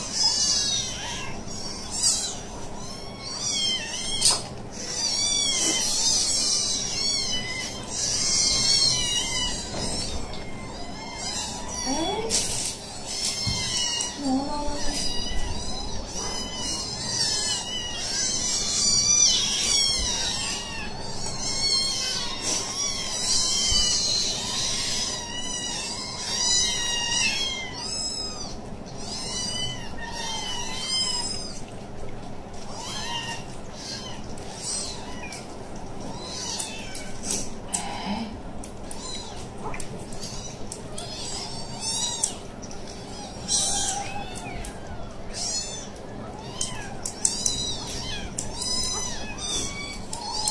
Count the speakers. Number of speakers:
0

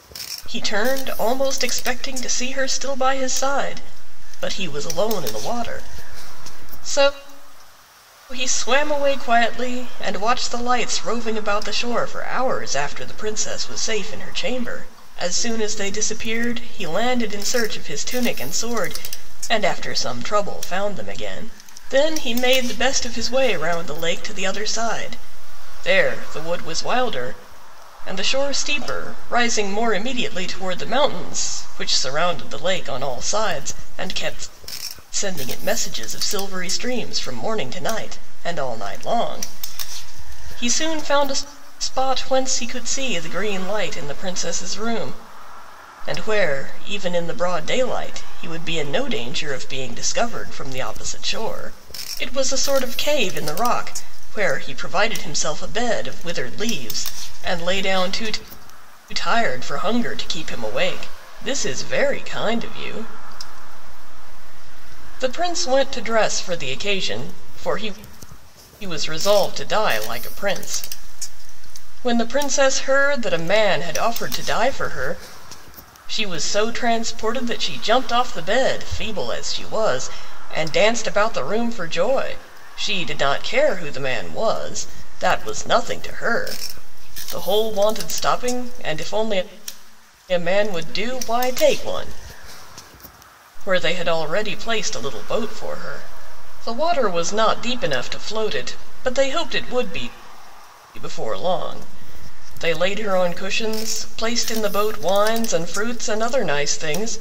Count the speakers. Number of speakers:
1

